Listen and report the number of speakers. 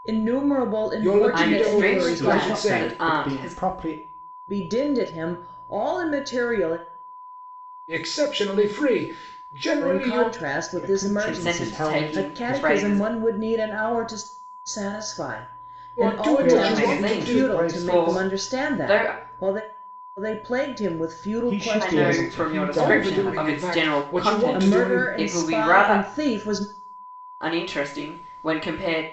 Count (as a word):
four